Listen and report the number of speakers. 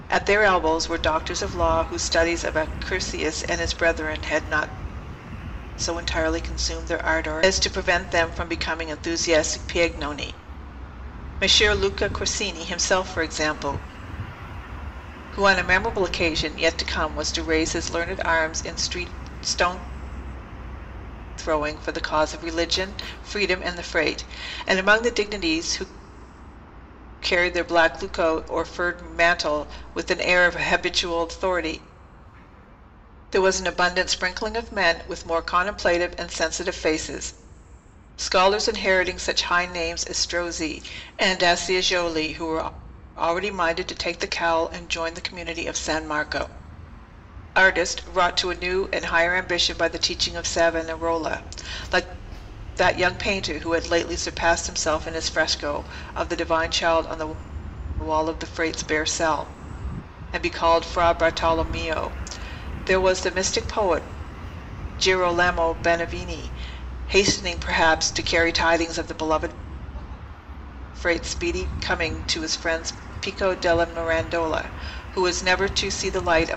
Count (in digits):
1